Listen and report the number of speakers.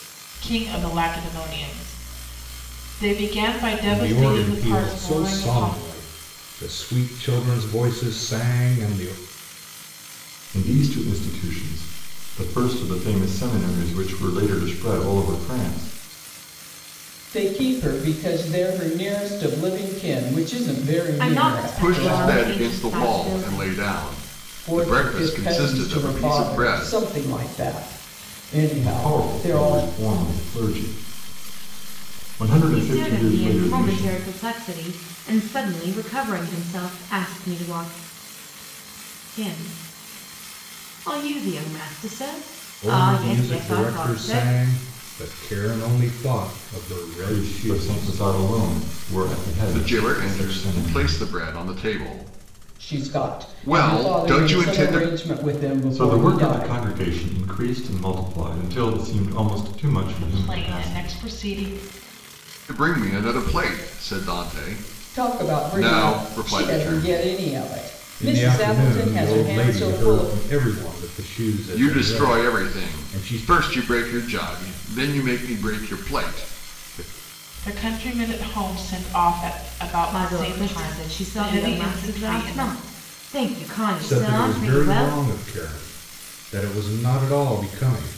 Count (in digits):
6